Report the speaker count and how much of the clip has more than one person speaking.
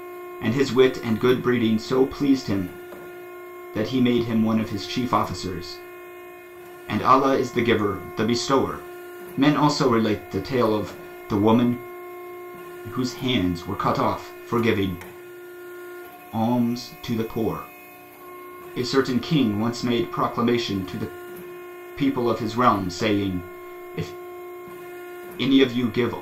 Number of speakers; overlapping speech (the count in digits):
1, no overlap